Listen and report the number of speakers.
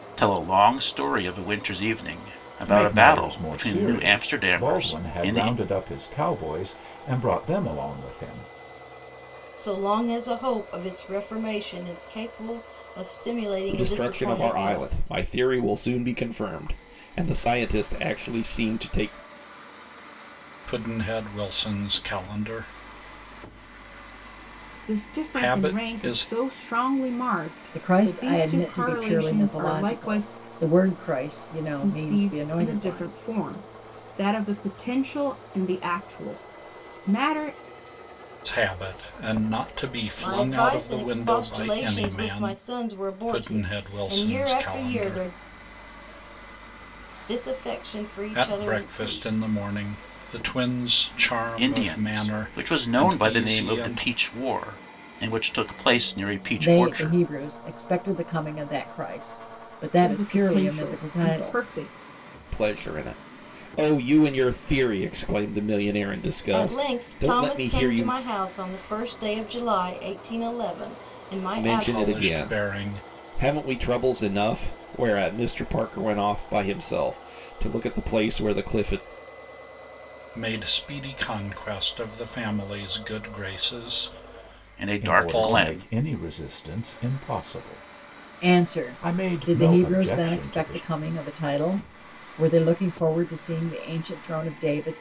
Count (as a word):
seven